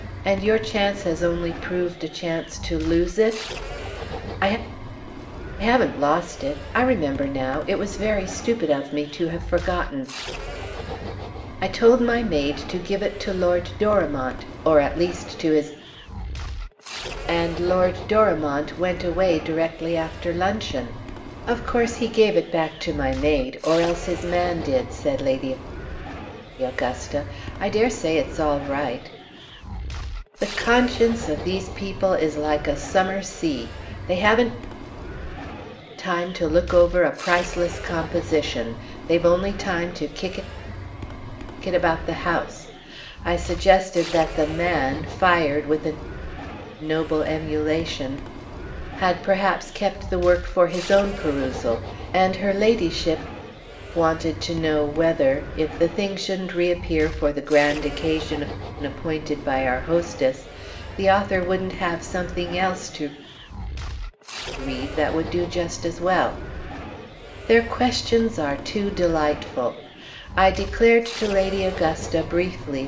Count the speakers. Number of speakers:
1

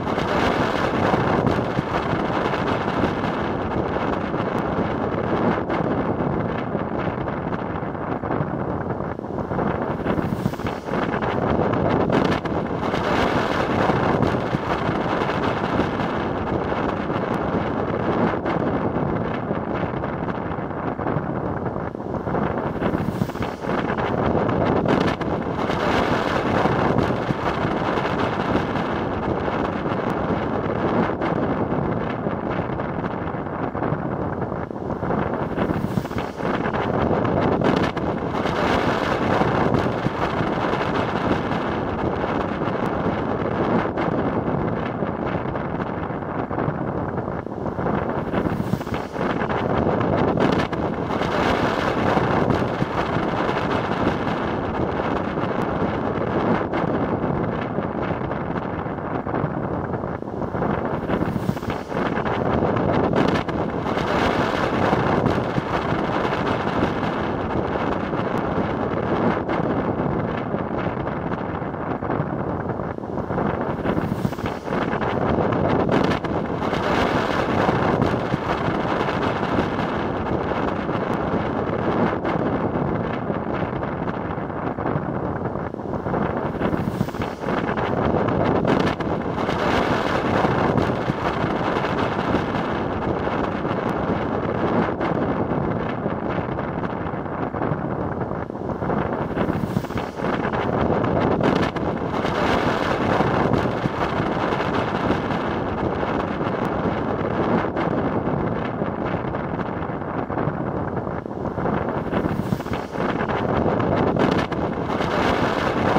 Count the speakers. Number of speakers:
0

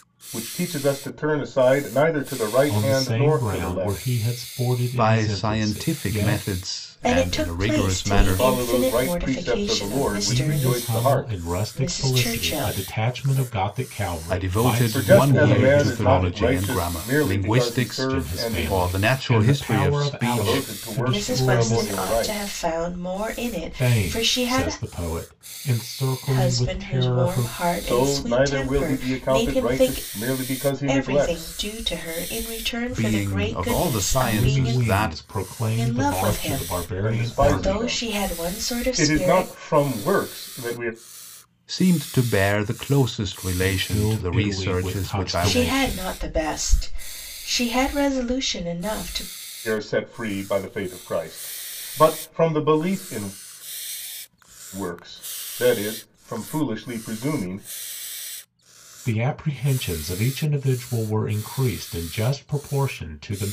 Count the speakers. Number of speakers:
4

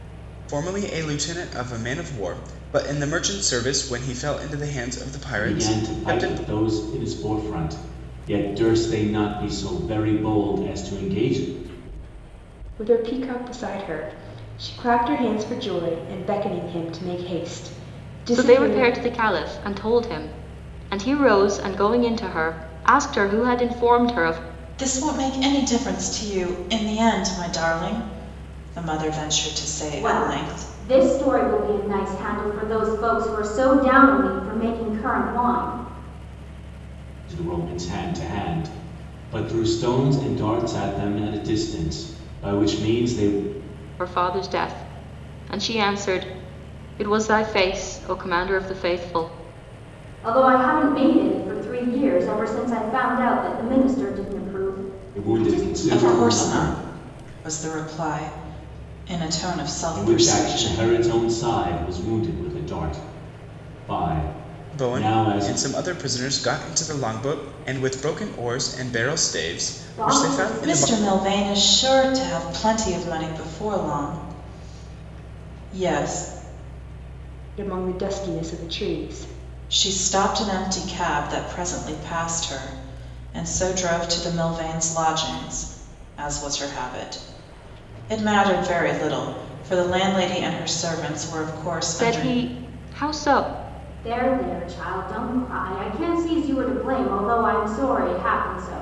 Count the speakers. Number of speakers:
6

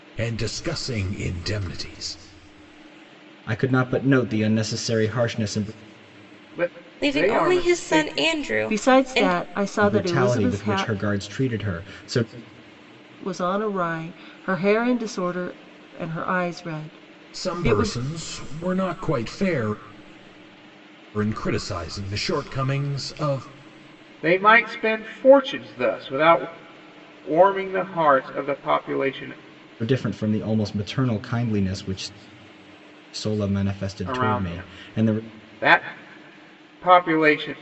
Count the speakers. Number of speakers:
5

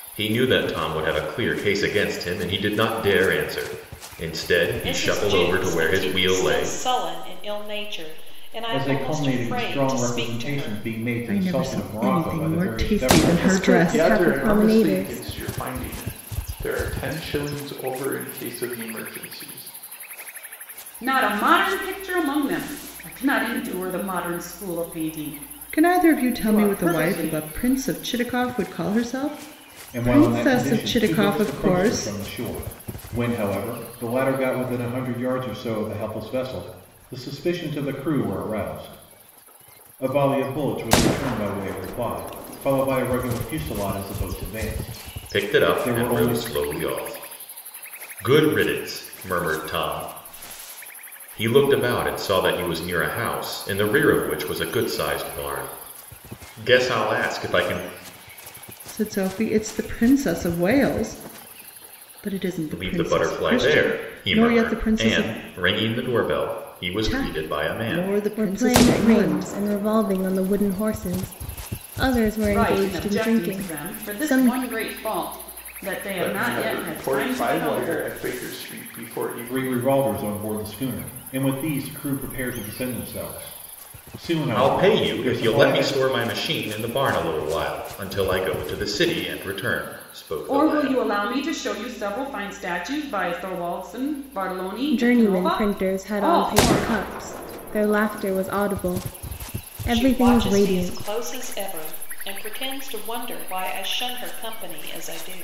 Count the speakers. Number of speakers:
7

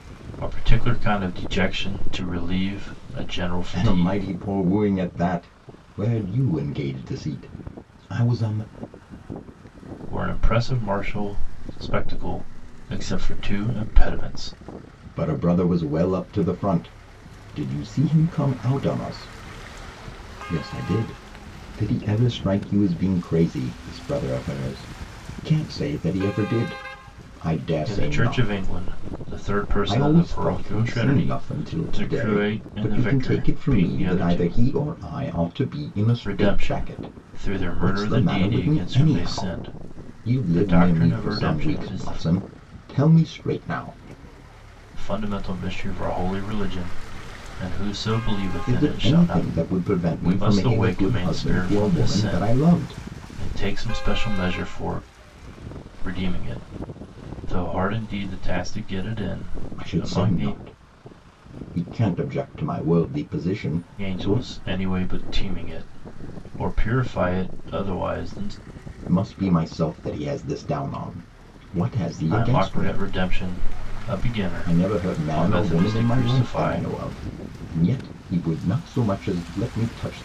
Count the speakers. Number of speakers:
2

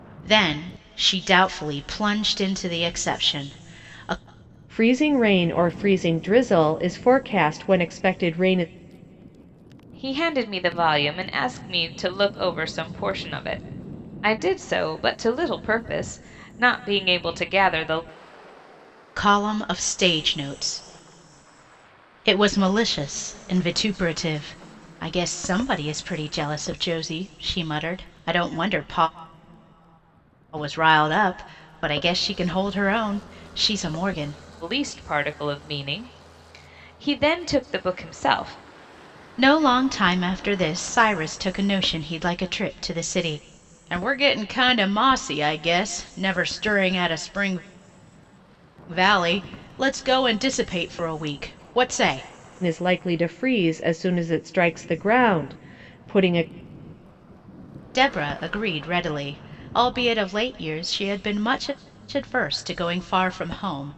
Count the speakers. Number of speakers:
3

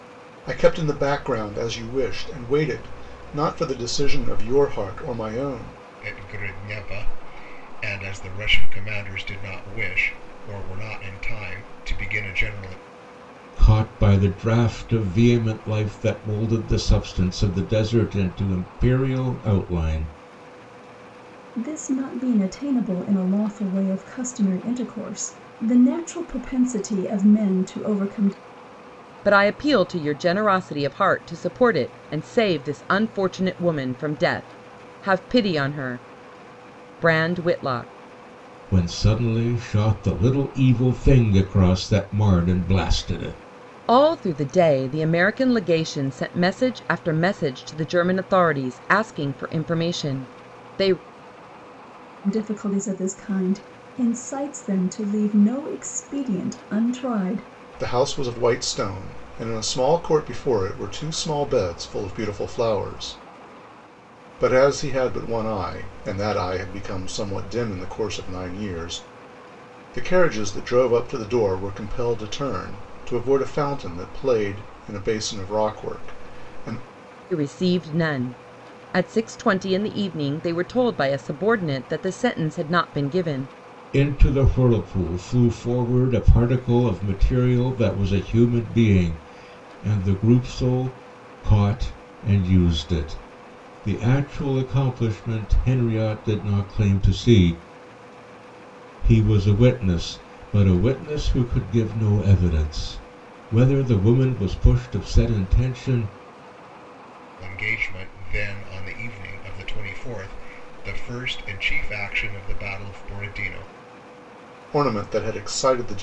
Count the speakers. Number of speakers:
5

